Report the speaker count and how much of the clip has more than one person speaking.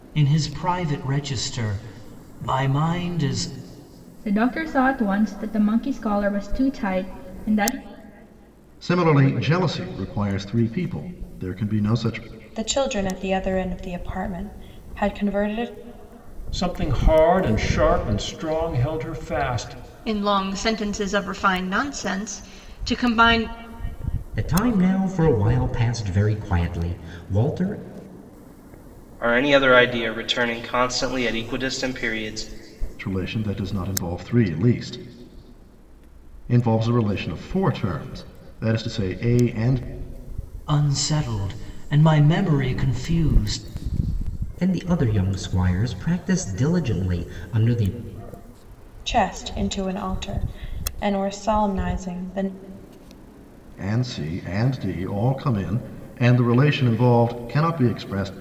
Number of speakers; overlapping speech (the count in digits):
8, no overlap